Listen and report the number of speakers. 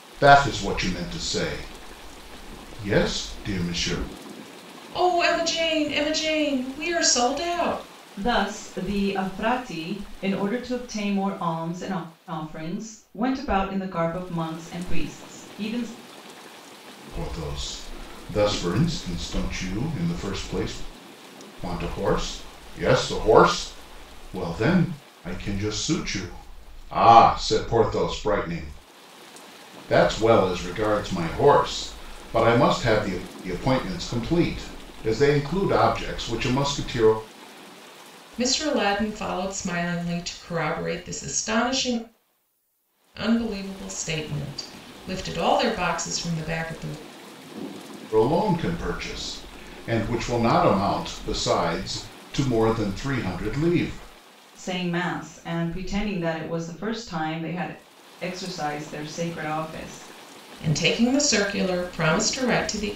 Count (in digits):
3